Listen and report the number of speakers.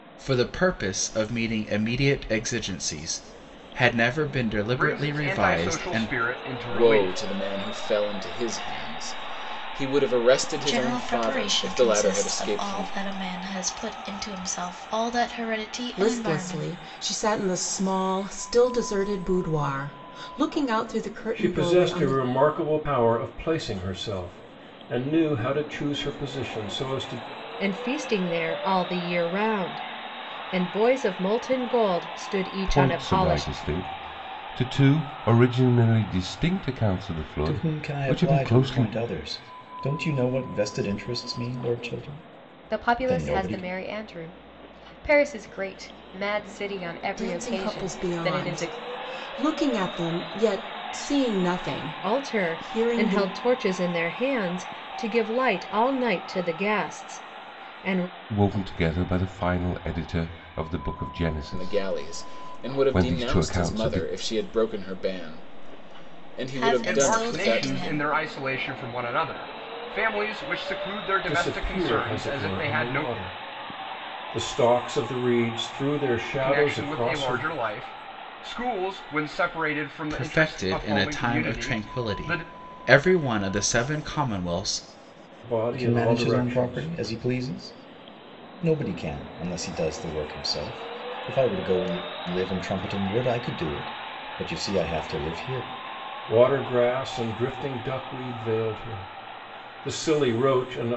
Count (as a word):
ten